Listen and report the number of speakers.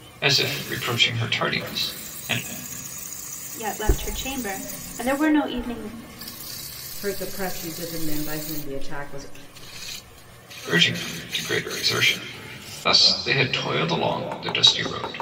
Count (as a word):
three